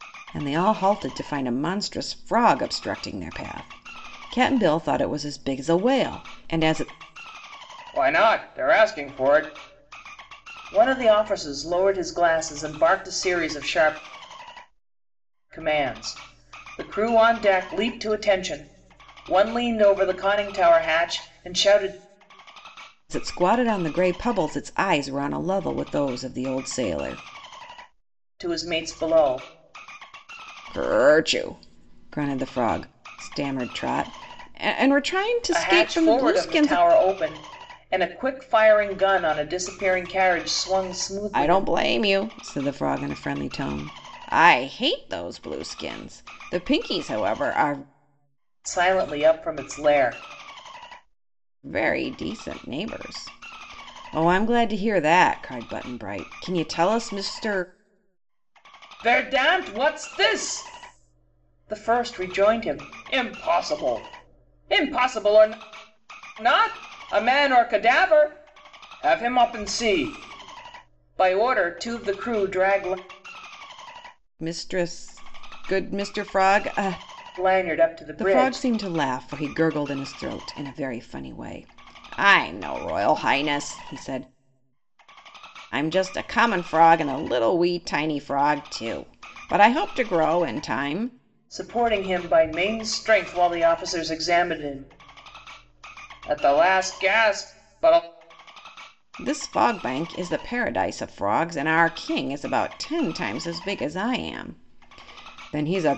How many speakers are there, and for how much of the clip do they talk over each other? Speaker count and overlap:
2, about 2%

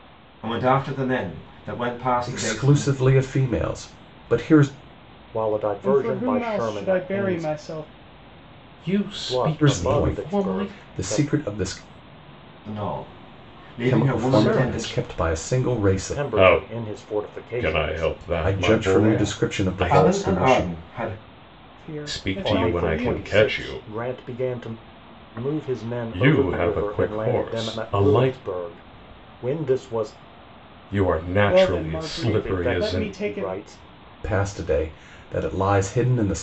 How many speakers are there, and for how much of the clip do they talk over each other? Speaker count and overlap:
5, about 46%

